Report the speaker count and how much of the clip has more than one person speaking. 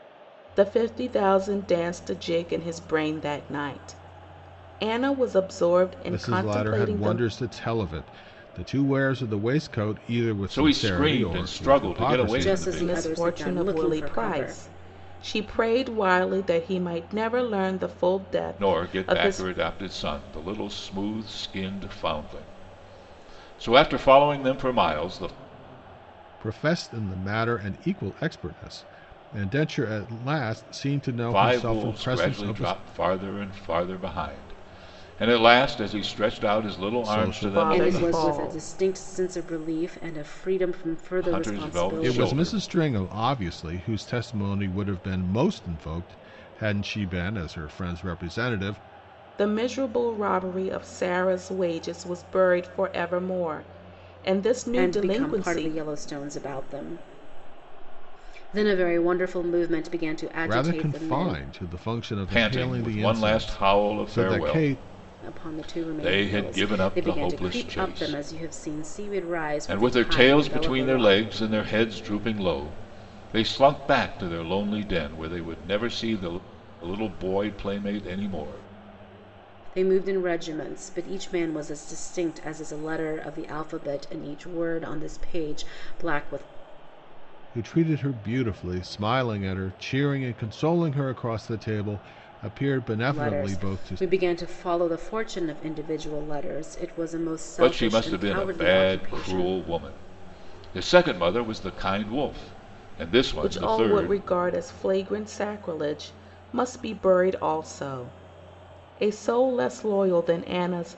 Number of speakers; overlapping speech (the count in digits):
4, about 21%